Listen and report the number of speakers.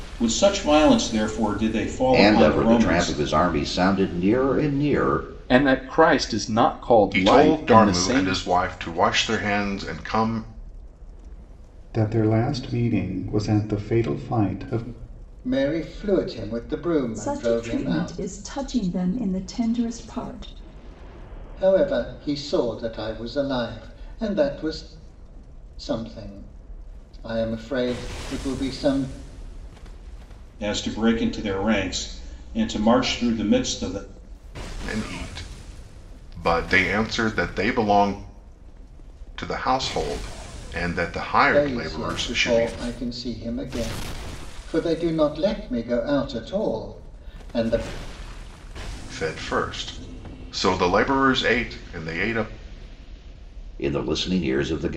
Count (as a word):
seven